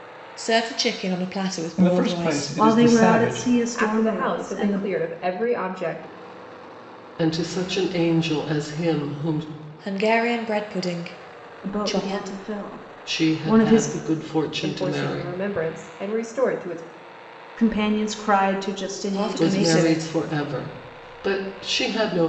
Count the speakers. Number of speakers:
5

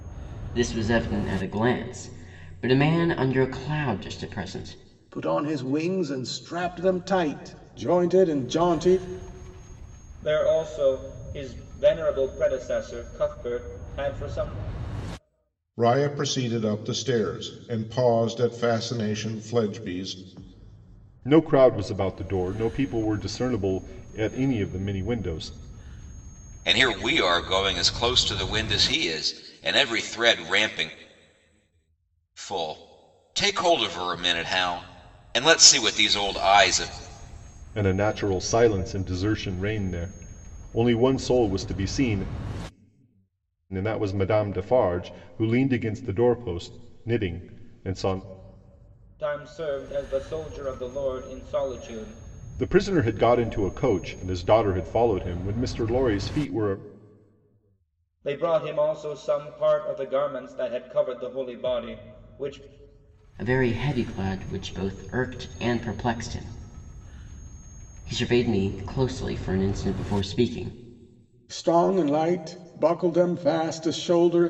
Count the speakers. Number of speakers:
6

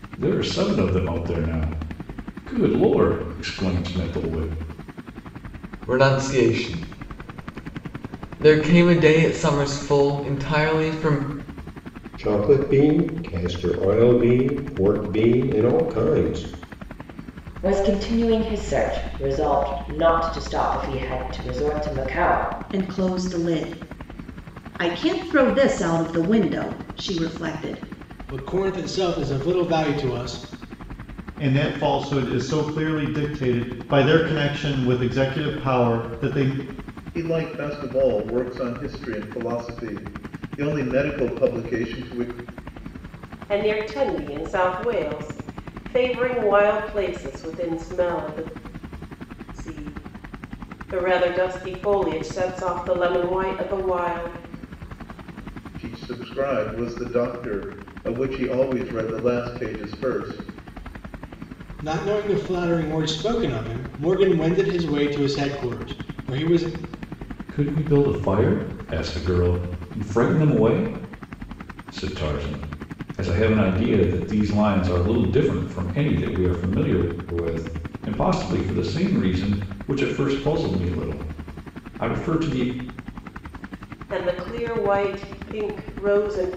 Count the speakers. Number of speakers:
9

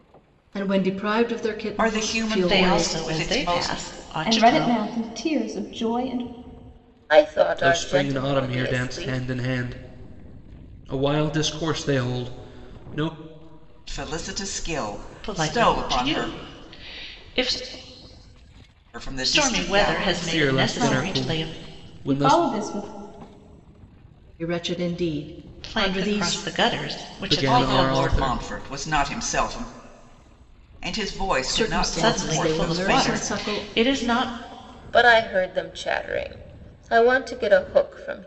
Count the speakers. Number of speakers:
6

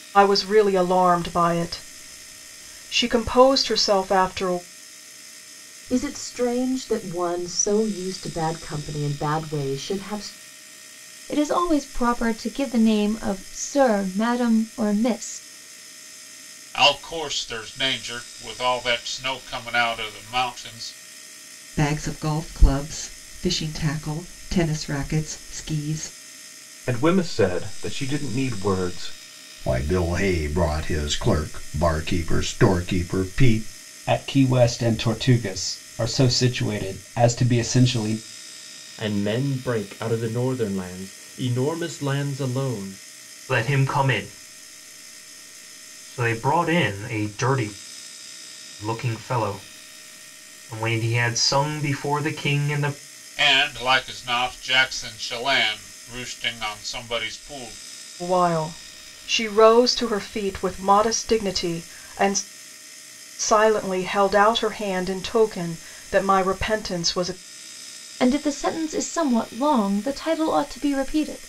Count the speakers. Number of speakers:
10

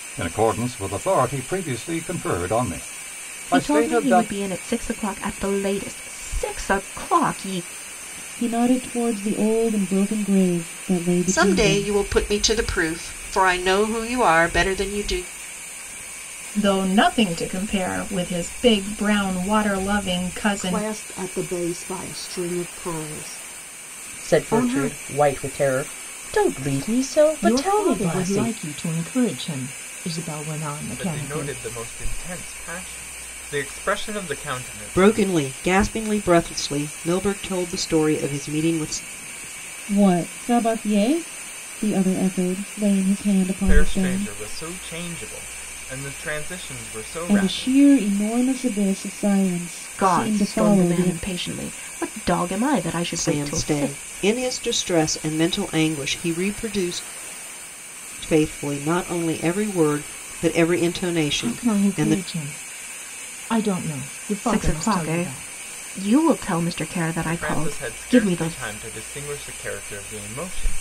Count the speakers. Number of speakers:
10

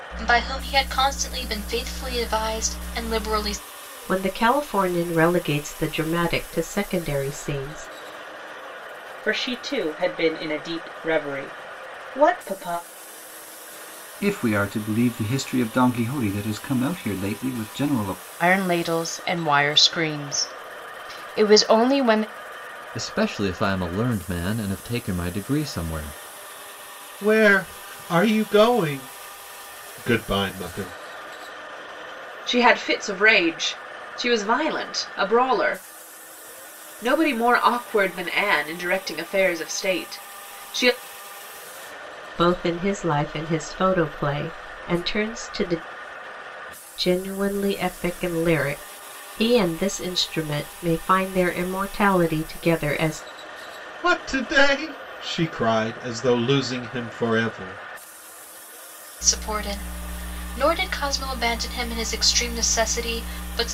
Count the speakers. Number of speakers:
8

